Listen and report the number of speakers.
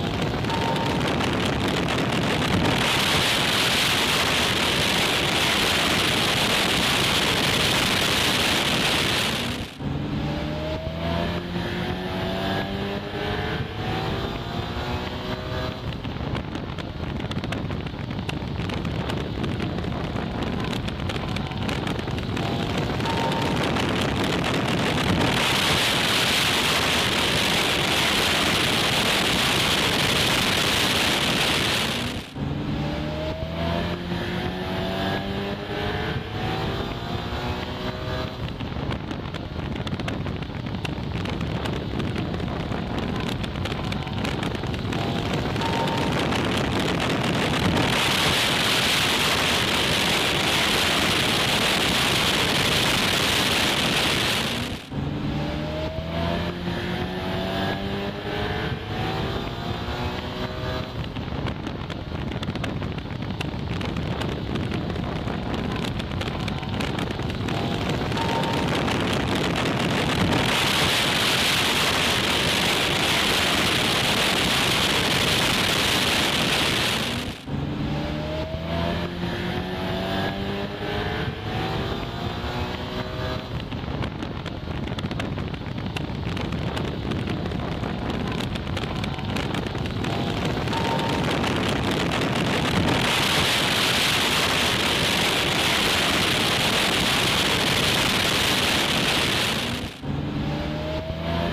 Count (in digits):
0